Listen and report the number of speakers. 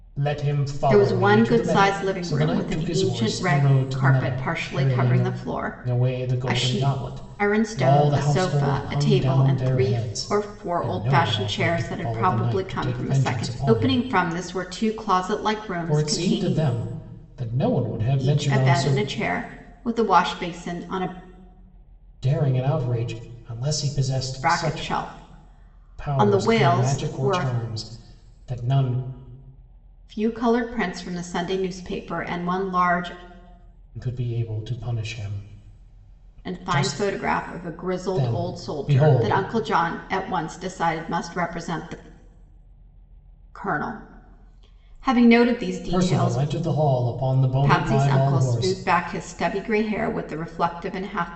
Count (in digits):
2